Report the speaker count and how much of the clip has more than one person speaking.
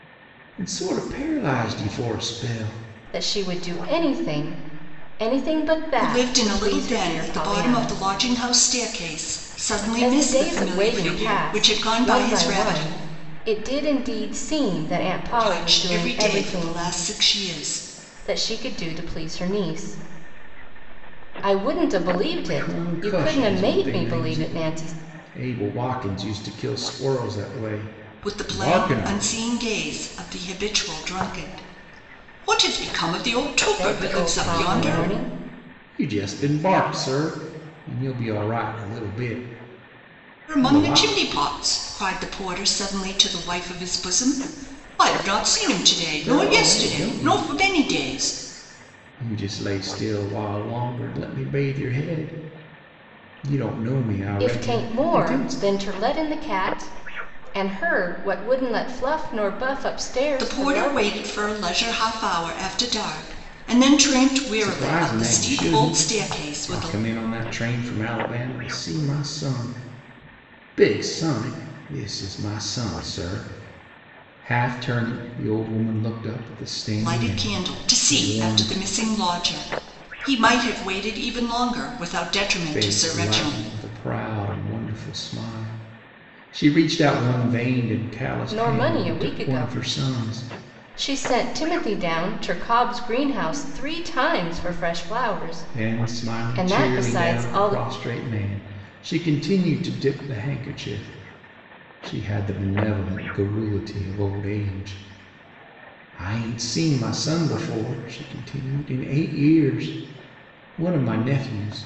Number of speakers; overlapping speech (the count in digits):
3, about 21%